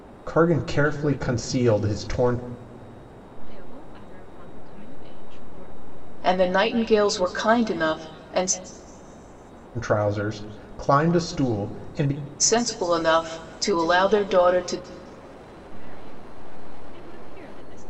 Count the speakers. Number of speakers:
three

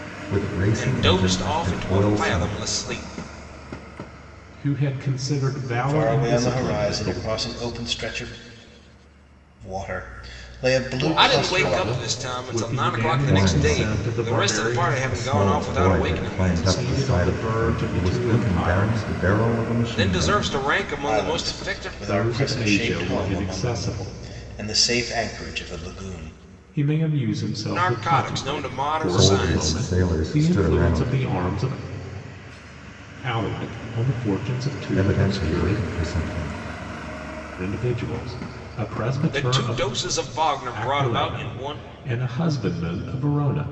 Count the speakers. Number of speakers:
four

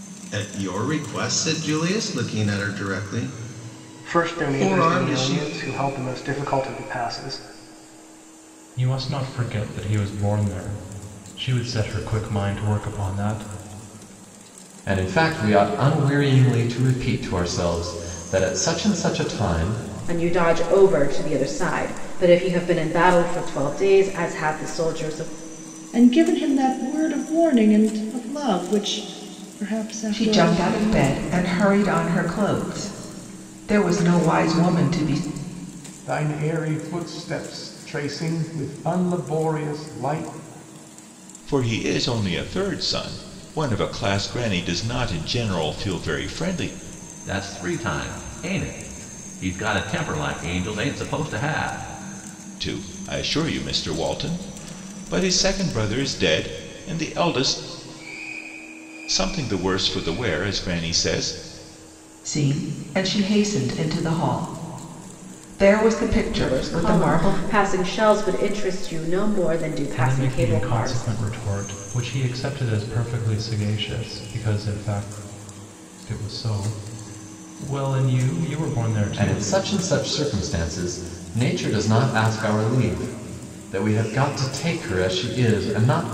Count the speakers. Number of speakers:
ten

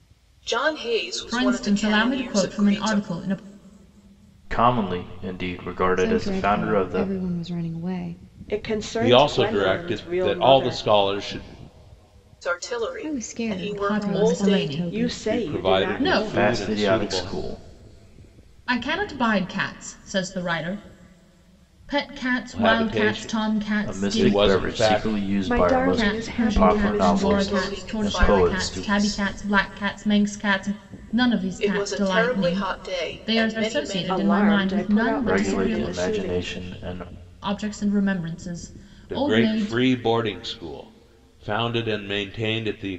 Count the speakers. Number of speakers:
six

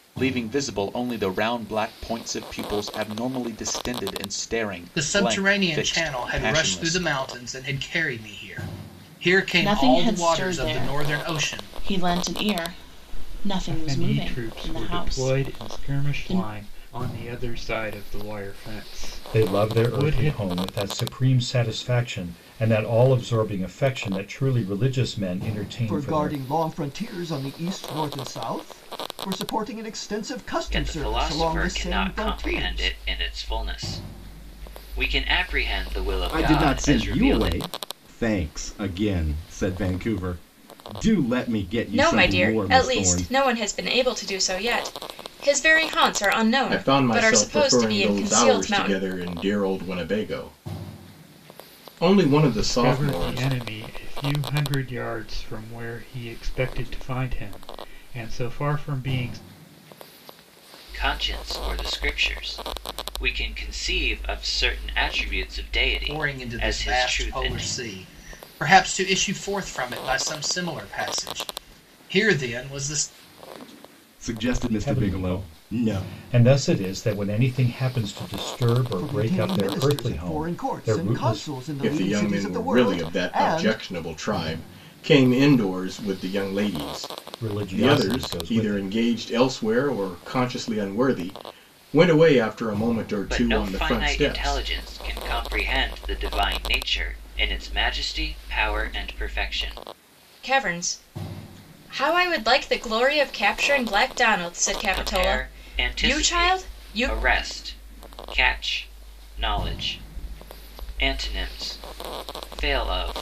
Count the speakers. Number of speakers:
ten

